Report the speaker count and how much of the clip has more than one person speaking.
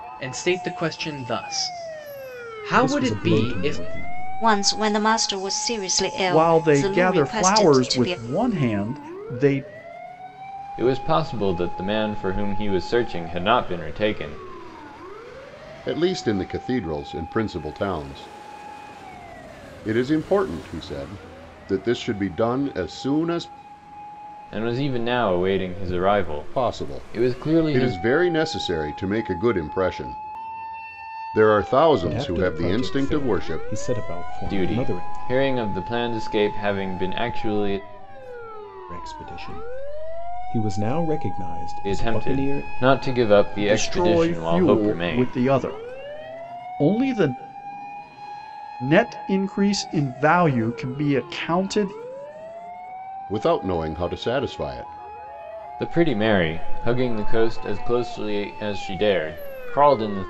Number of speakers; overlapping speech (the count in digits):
6, about 16%